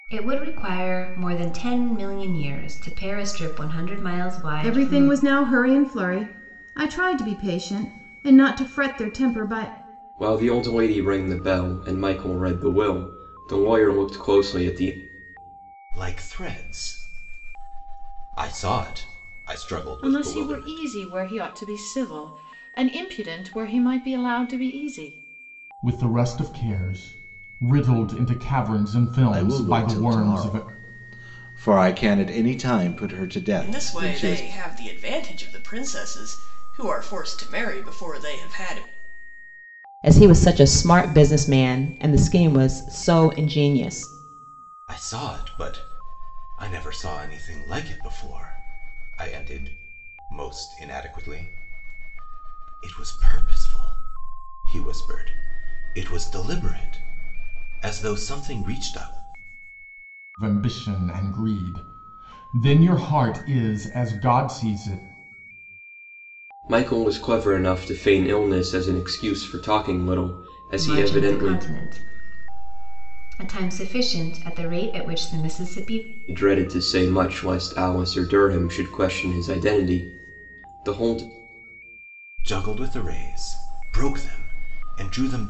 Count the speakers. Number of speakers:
nine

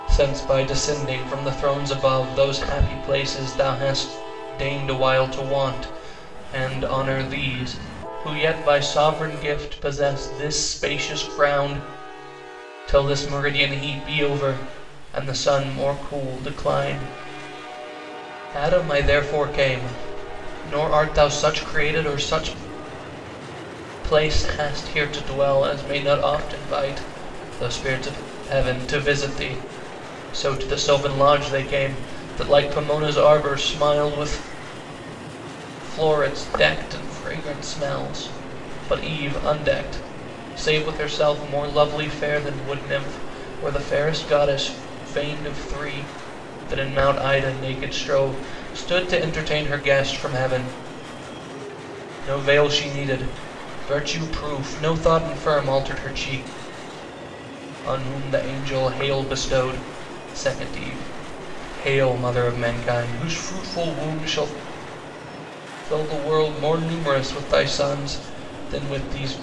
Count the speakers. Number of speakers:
one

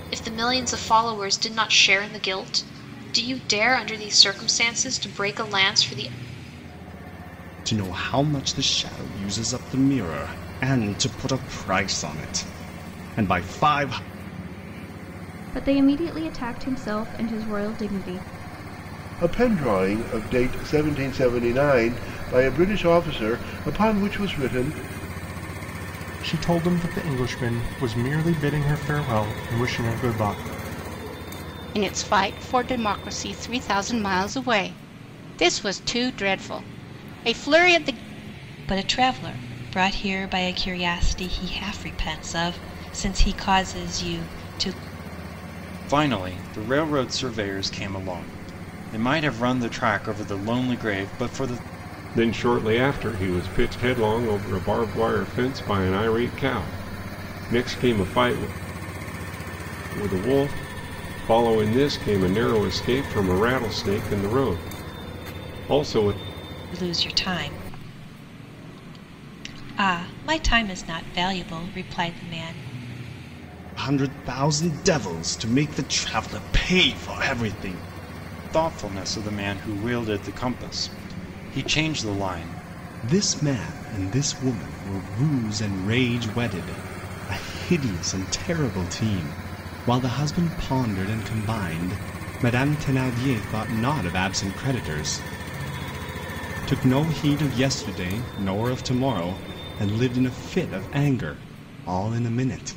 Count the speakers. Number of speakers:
nine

